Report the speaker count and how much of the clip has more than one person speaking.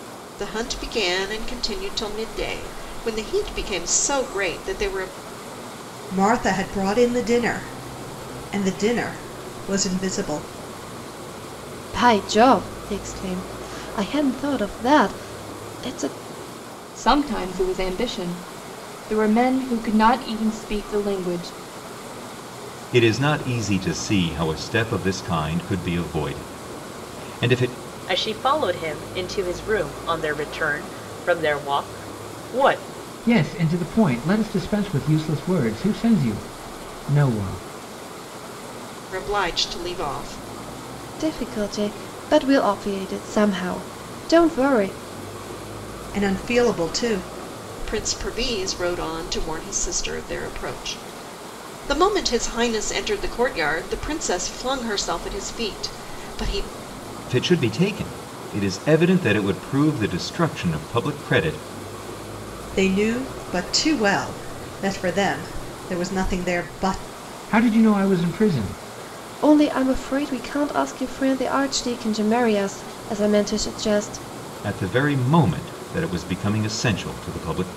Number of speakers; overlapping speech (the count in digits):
7, no overlap